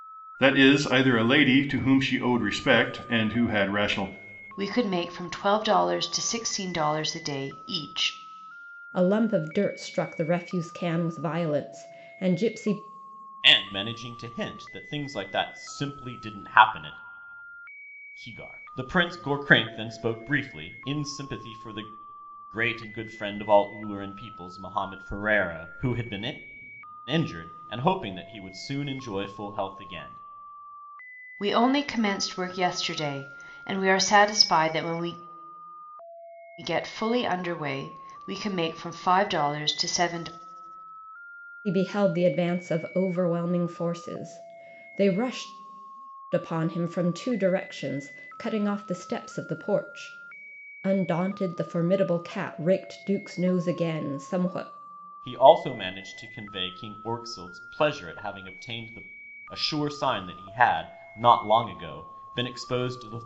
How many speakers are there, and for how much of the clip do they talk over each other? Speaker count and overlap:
four, no overlap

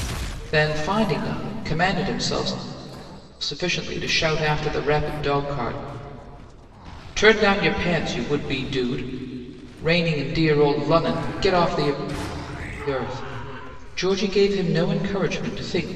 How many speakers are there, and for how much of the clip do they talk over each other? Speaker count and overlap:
one, no overlap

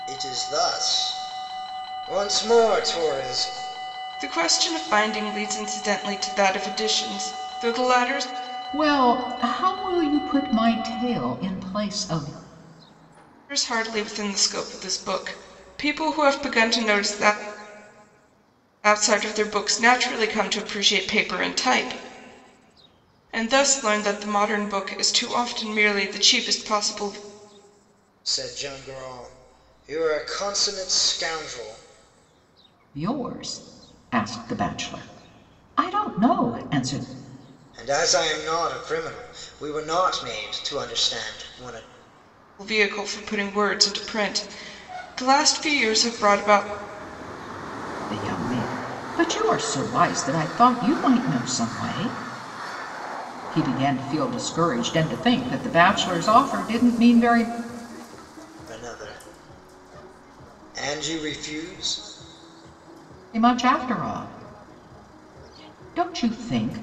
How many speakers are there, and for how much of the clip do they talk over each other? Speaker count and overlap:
three, no overlap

